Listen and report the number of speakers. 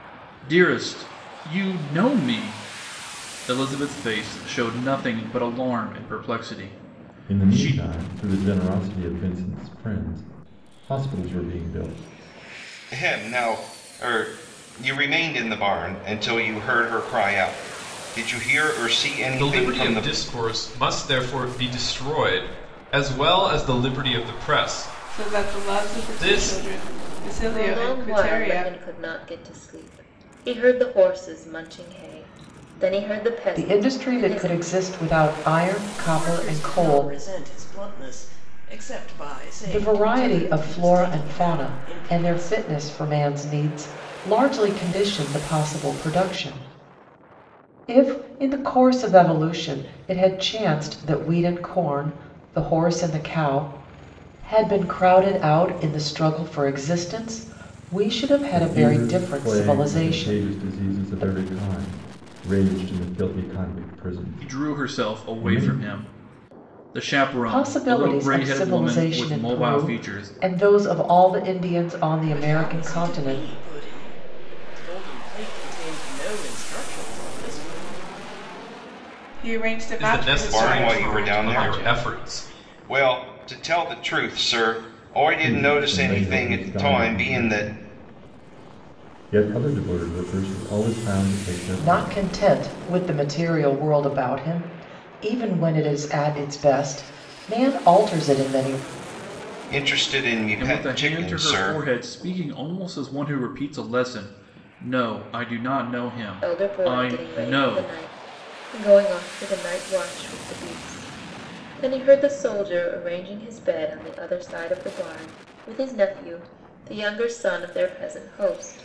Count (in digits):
8